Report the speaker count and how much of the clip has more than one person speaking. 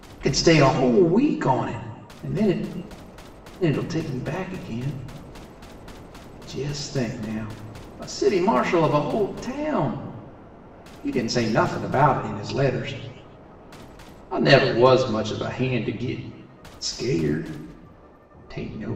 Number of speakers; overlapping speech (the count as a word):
one, no overlap